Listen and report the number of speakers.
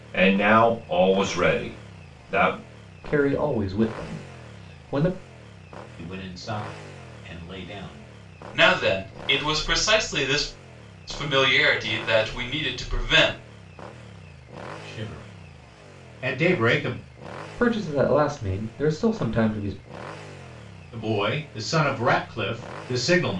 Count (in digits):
4